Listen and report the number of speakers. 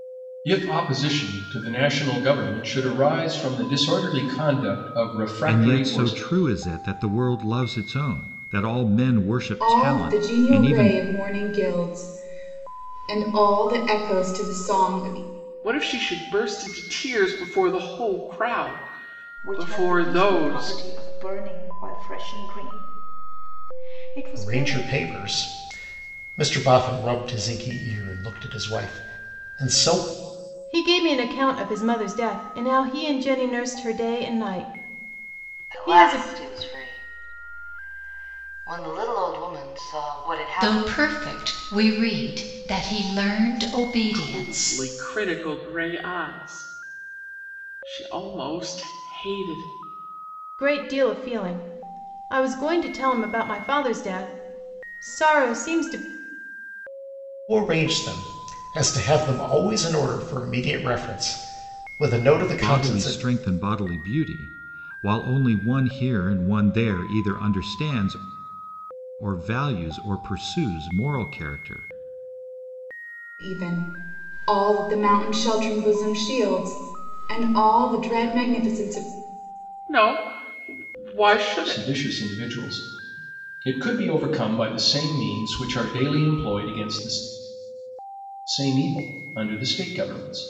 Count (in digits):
9